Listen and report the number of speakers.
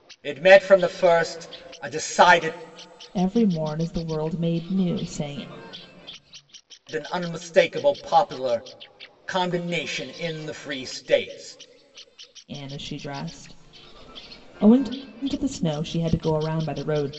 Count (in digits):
2